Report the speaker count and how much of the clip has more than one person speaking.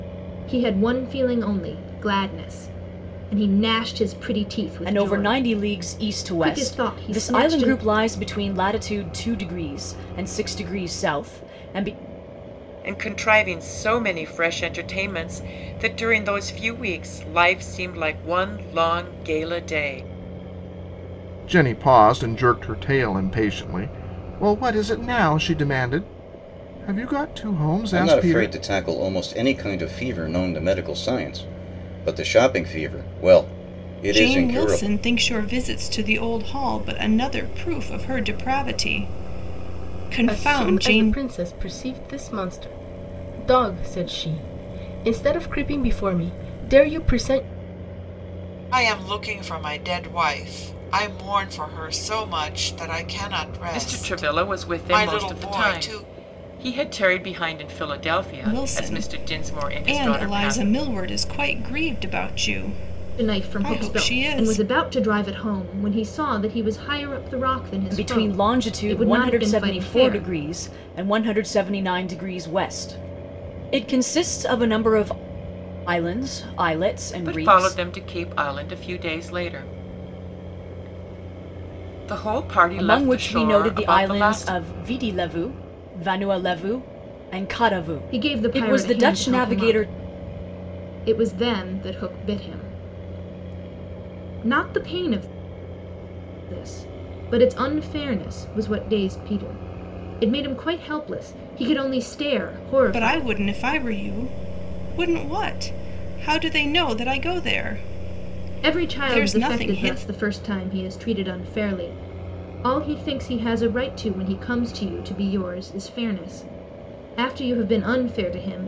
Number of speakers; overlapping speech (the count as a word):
eight, about 17%